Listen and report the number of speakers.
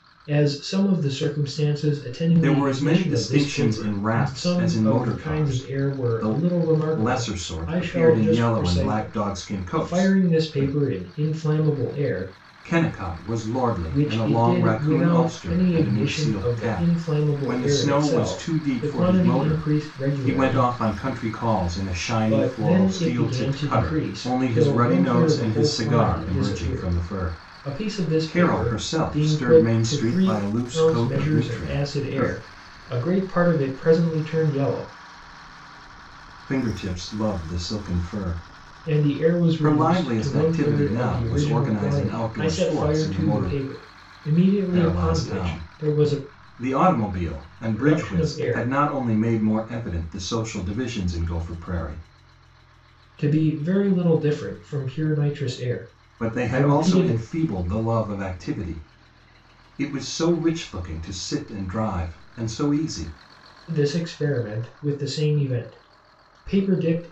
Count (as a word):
two